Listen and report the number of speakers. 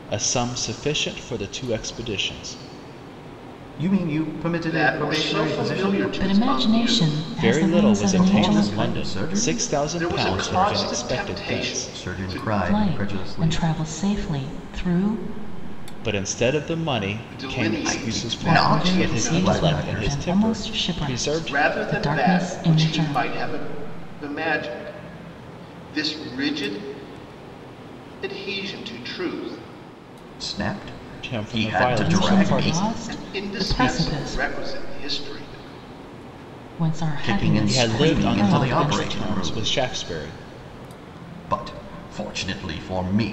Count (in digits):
4